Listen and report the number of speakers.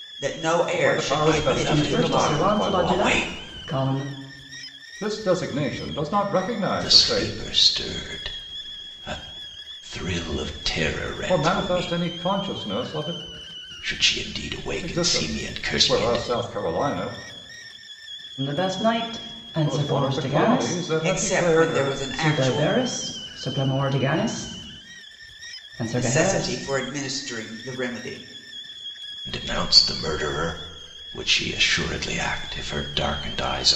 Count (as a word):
four